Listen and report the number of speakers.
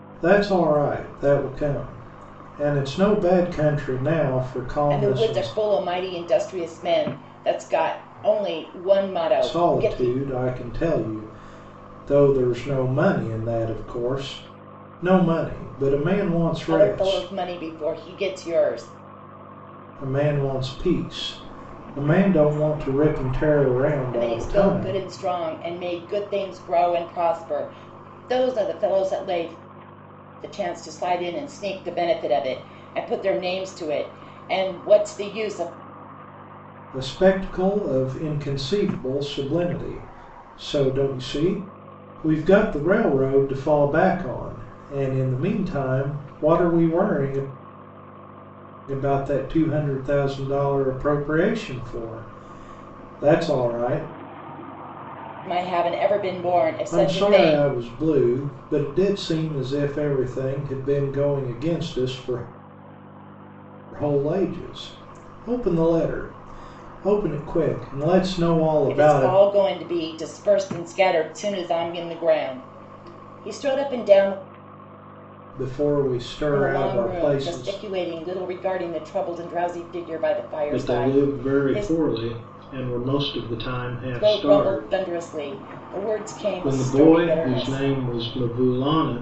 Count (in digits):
2